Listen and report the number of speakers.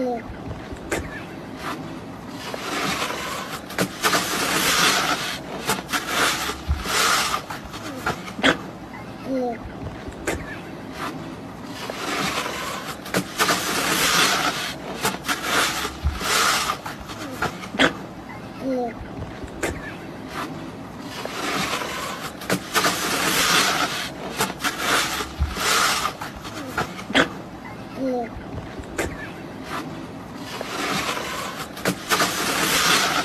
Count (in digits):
0